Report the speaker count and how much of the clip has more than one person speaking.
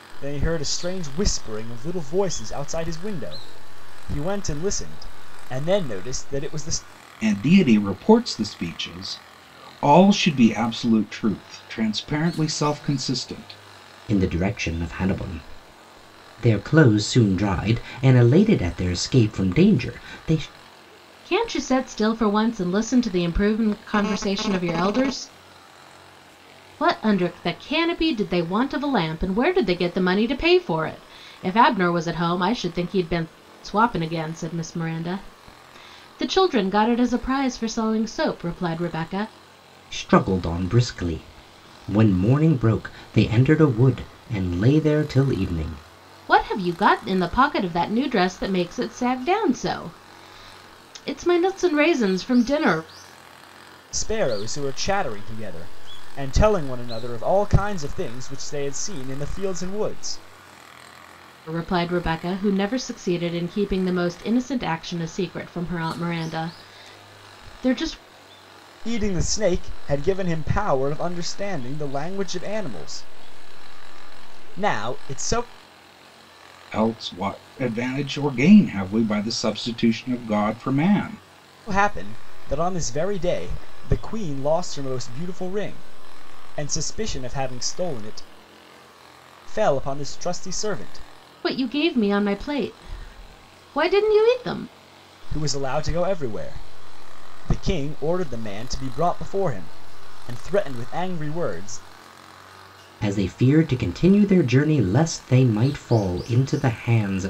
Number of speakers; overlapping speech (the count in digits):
4, no overlap